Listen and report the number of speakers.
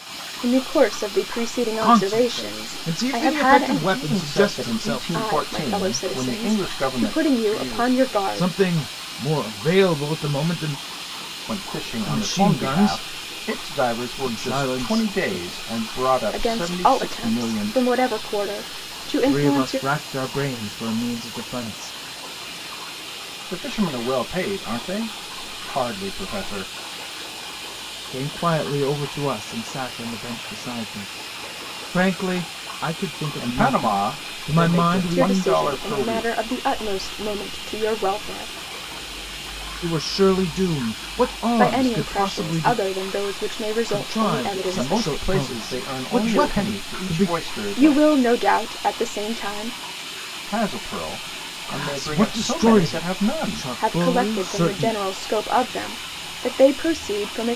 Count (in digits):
3